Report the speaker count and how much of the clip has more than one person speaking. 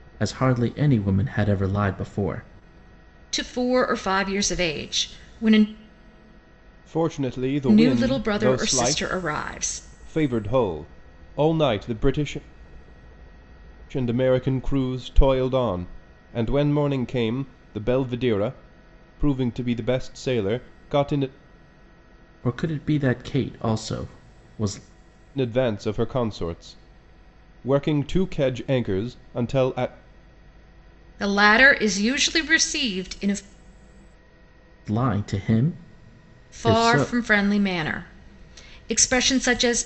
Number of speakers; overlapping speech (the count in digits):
3, about 5%